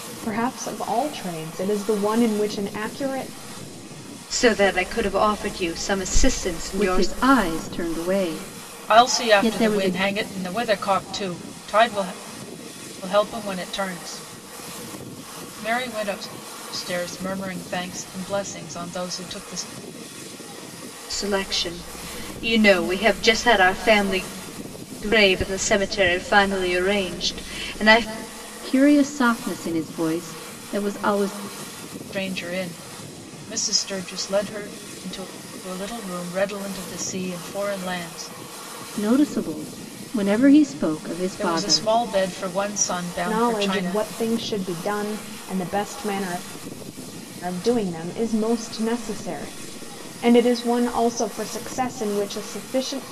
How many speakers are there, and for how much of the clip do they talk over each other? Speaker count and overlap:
four, about 5%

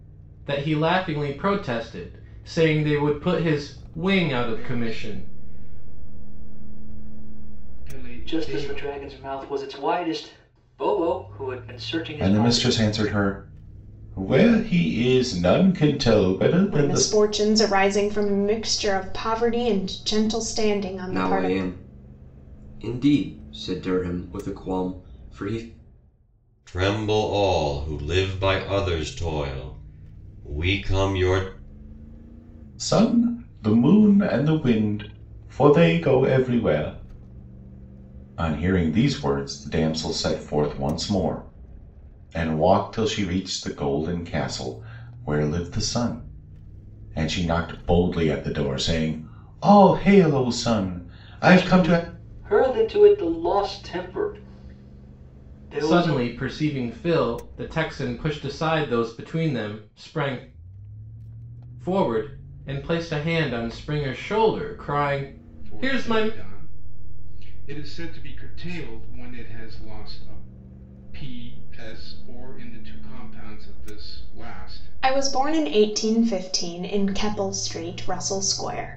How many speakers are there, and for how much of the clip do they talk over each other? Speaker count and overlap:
seven, about 7%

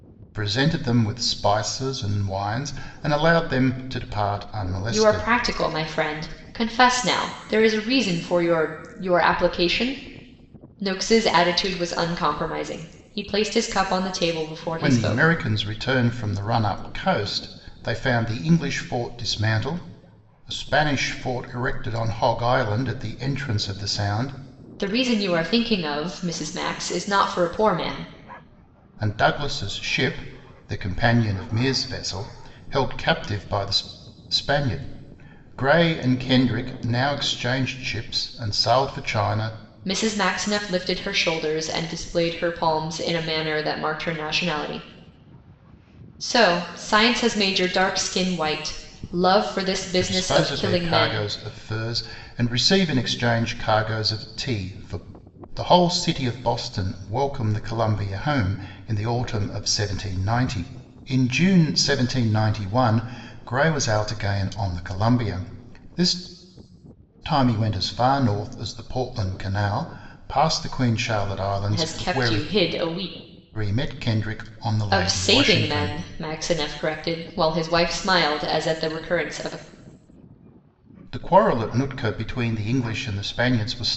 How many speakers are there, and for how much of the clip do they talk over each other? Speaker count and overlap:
two, about 5%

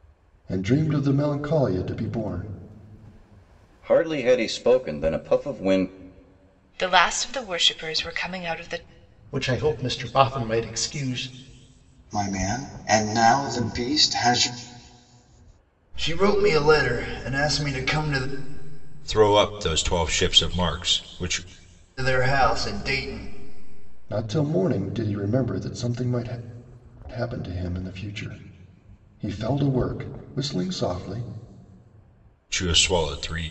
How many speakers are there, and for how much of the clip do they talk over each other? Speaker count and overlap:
seven, no overlap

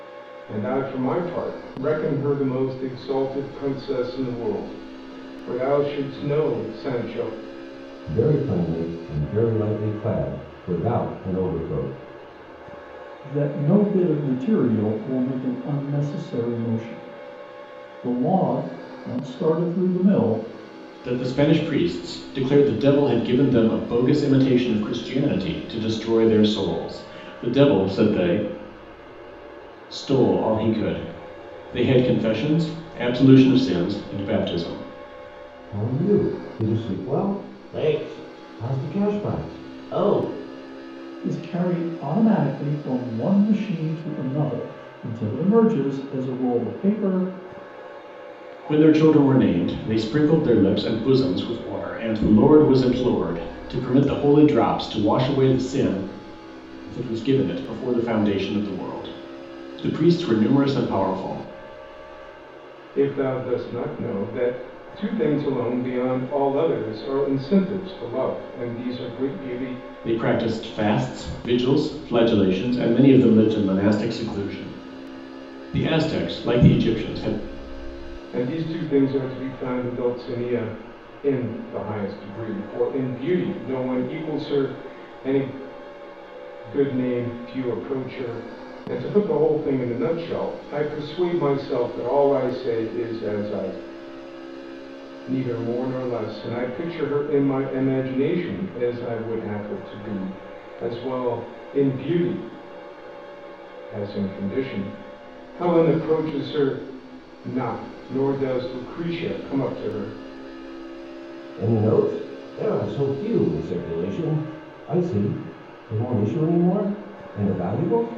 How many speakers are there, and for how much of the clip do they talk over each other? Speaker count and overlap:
four, no overlap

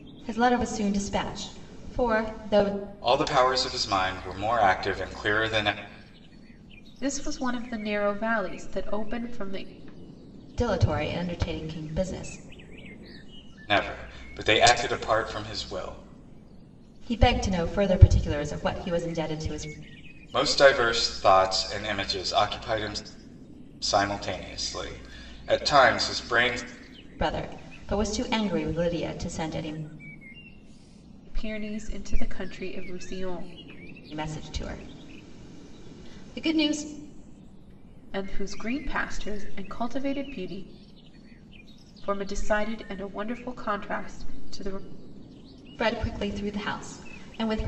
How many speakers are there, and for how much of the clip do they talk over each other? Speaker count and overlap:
three, no overlap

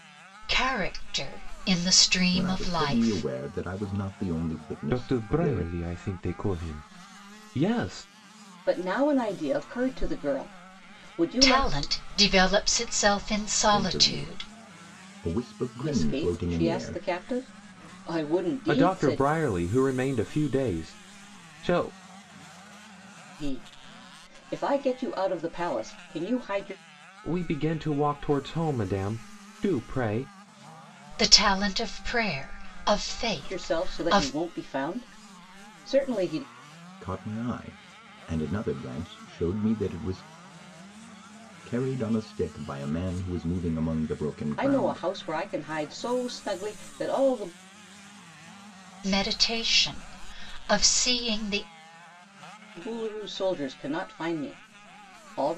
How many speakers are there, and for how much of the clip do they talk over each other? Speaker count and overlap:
four, about 12%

